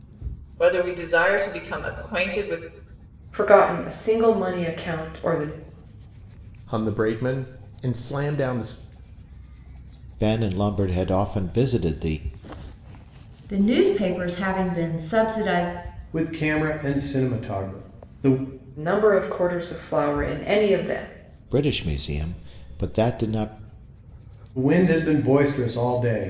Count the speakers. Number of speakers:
six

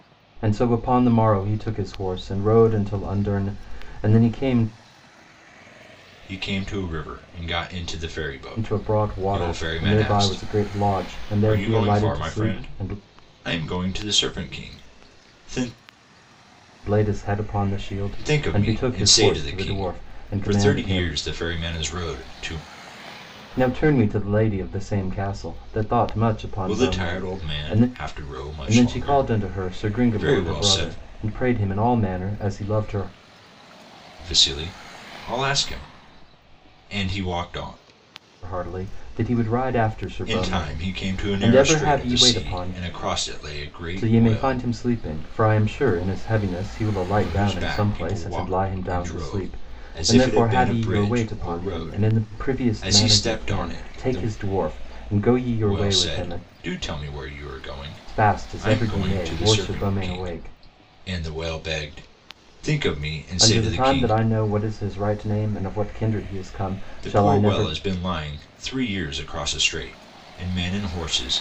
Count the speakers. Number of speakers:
two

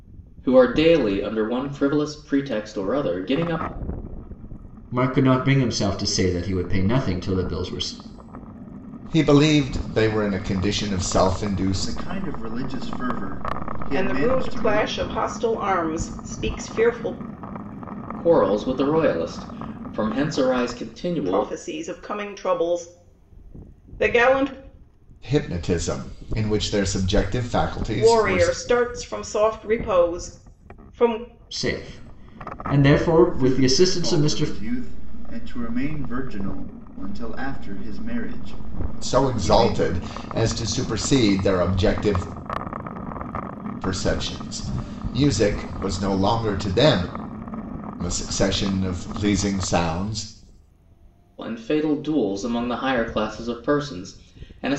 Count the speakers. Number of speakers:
five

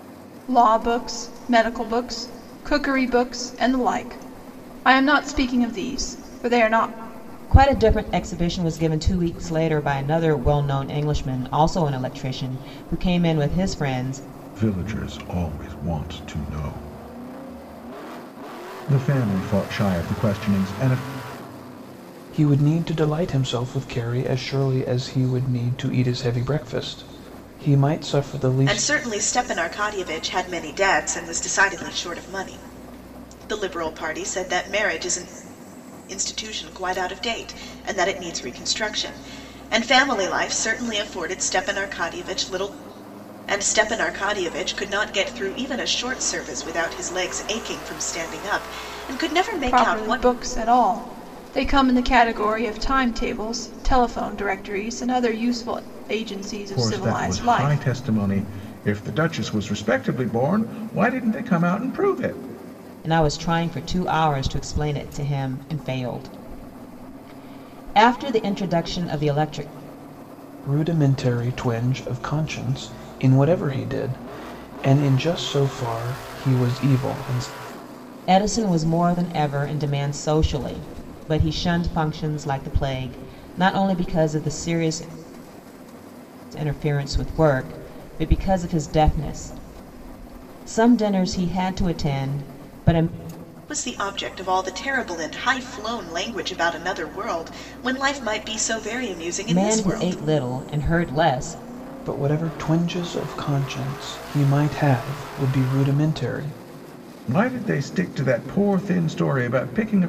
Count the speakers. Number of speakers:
five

